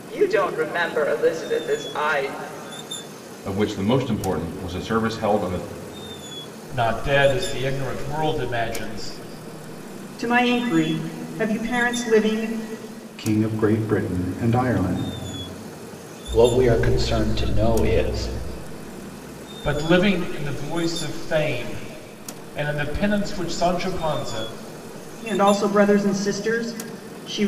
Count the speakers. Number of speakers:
six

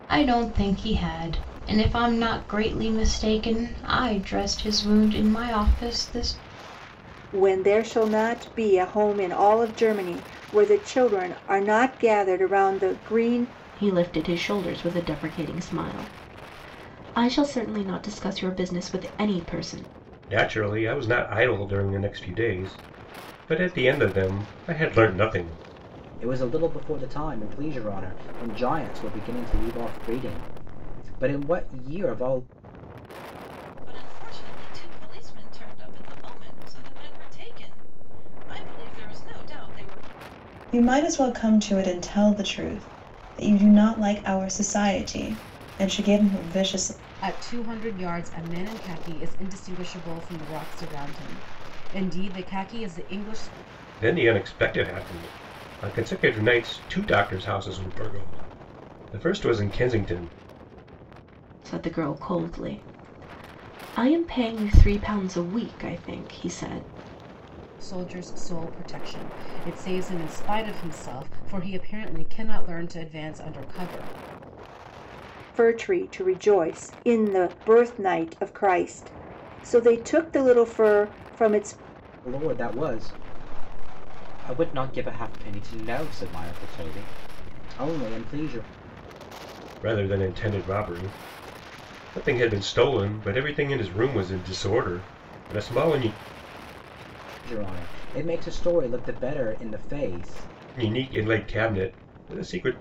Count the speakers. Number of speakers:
eight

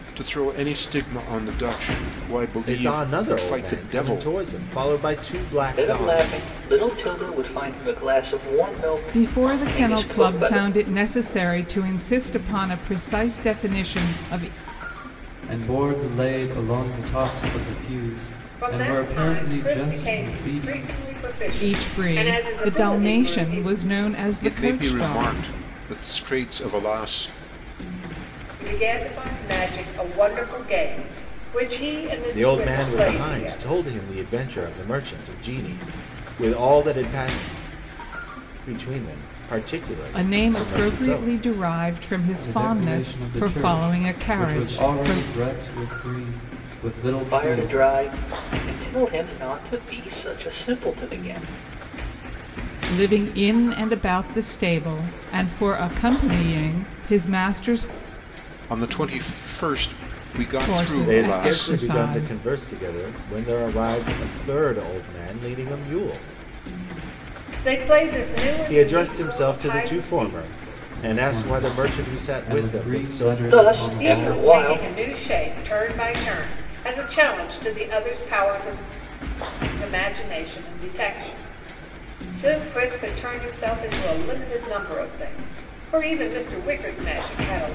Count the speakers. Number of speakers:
six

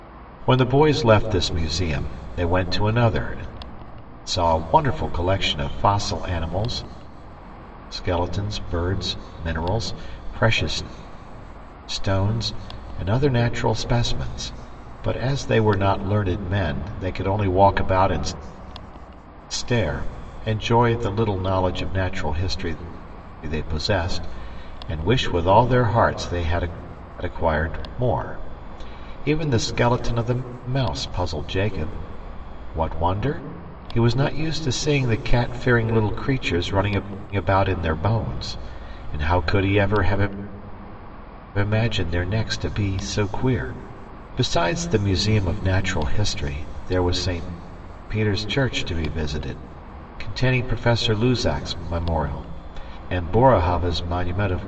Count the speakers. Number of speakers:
one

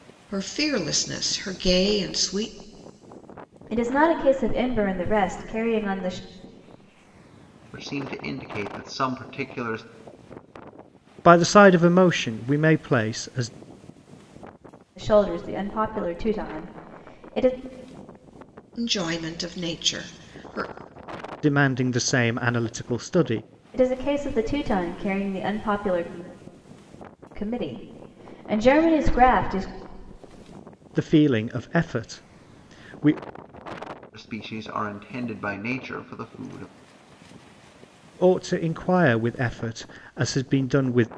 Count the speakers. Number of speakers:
four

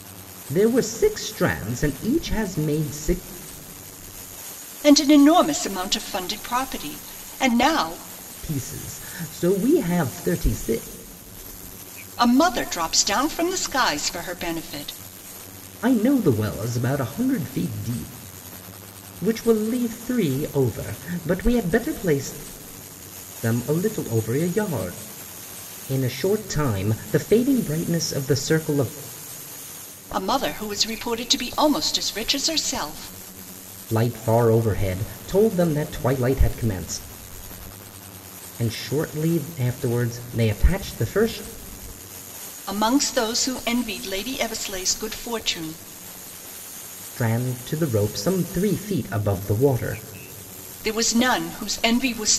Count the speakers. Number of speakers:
two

